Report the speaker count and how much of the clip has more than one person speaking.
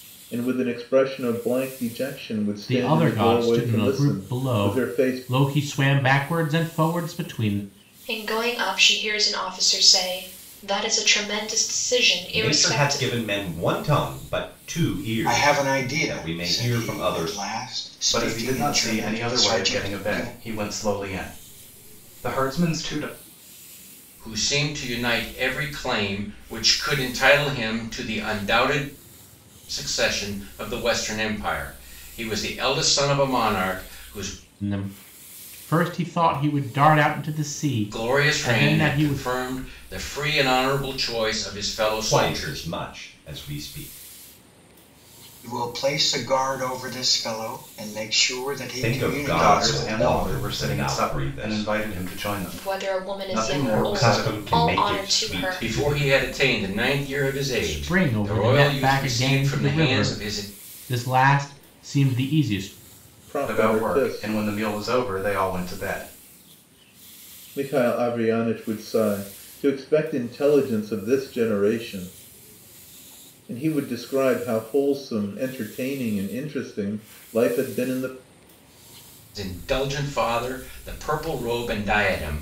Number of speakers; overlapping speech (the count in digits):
7, about 25%